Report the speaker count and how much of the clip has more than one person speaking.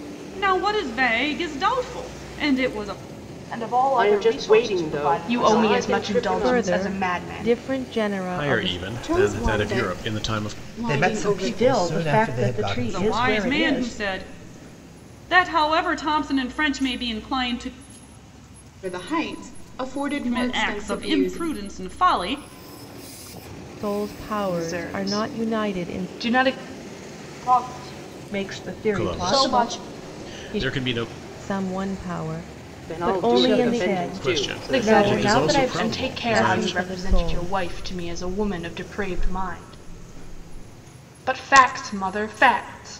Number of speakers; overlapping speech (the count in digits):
9, about 44%